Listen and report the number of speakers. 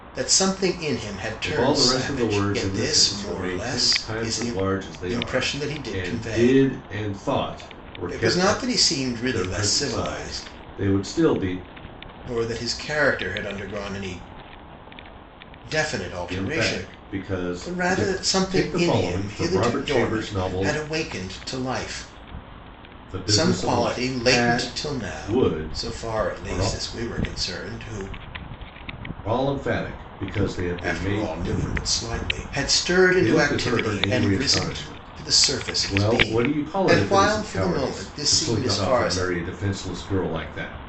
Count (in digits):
2